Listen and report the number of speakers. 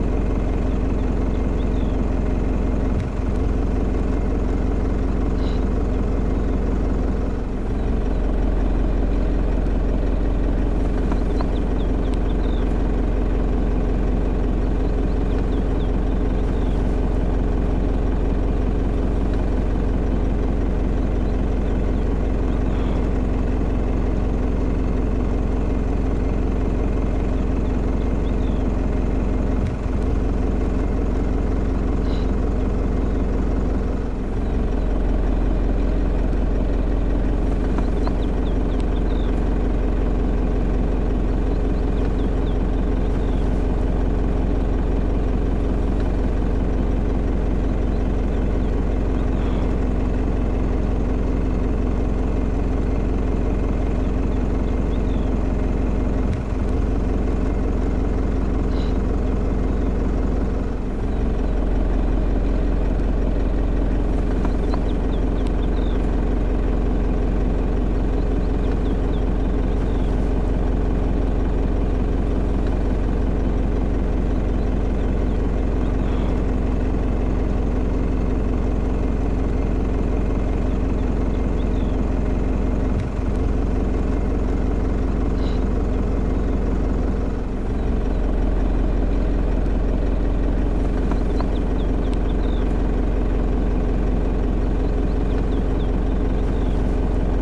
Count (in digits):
0